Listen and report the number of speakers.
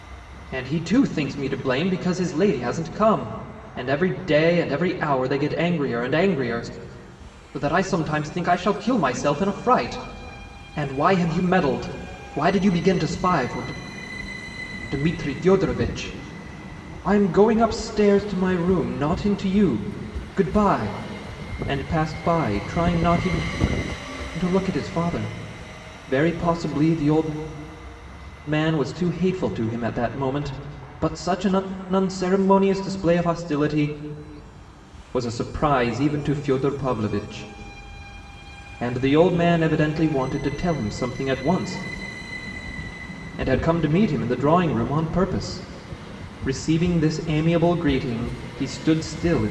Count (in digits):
1